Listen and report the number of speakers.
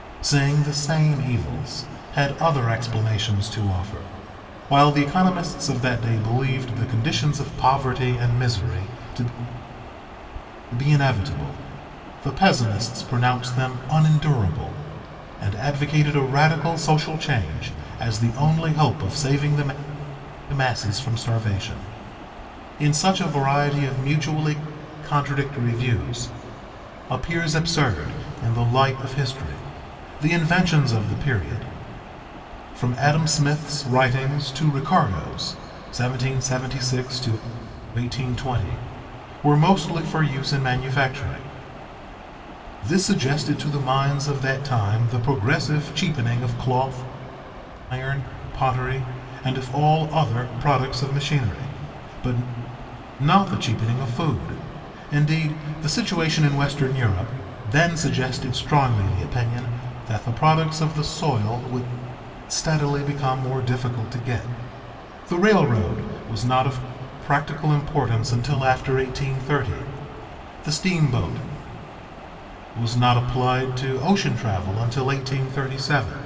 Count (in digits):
1